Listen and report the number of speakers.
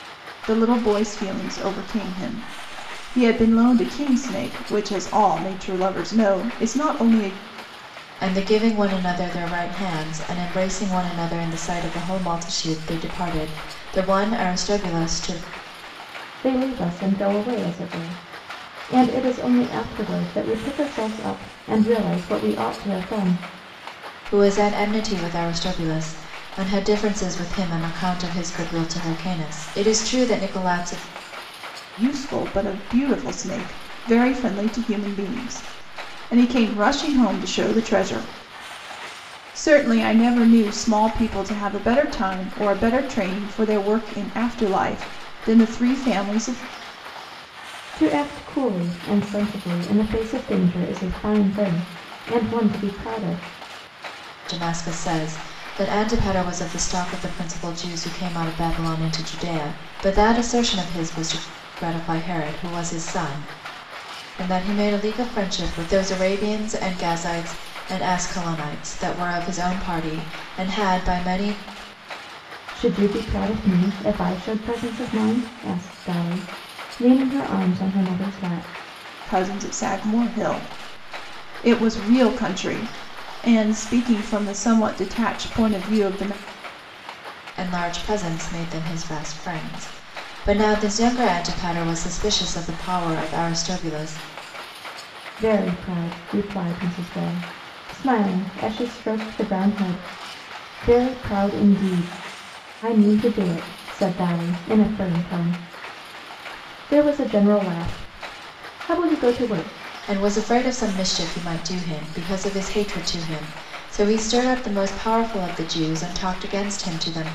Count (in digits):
3